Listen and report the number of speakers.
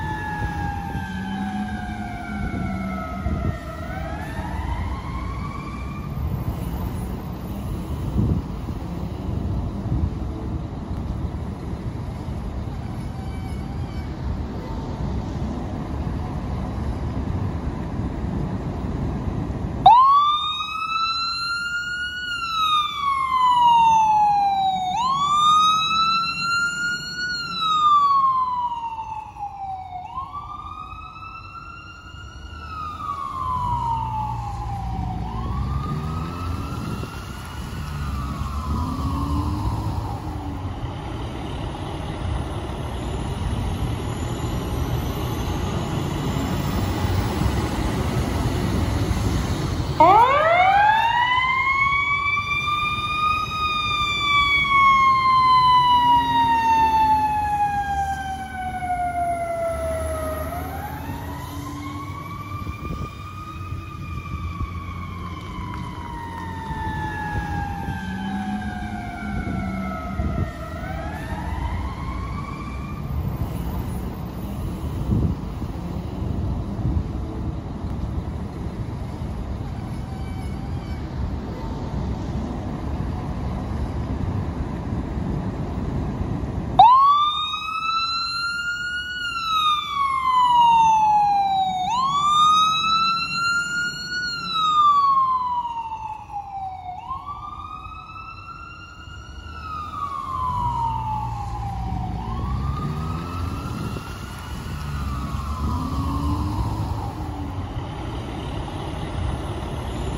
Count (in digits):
0